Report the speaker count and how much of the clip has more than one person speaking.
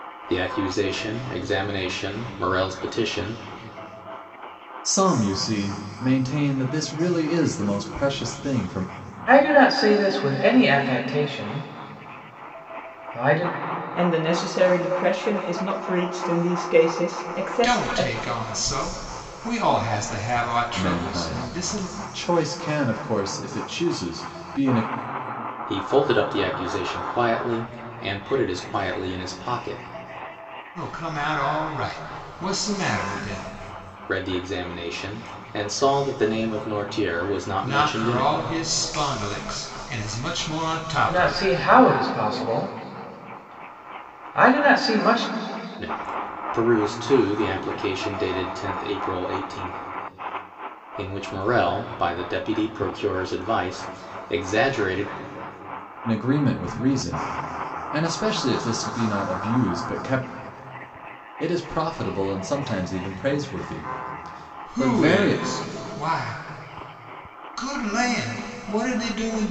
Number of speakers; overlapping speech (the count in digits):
5, about 5%